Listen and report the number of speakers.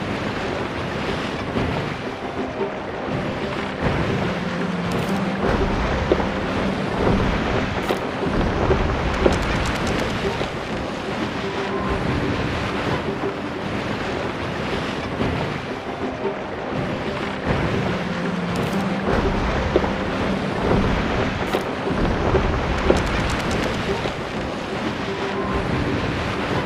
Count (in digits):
0